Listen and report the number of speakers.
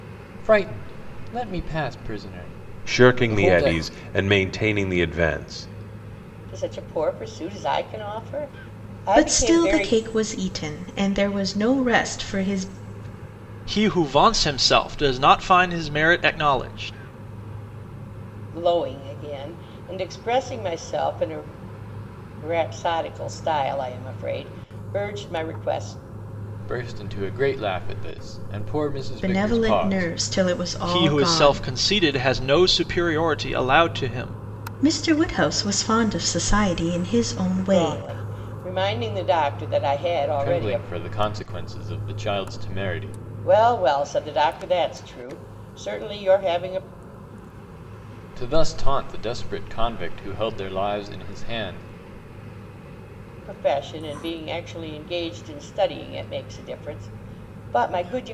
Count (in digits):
5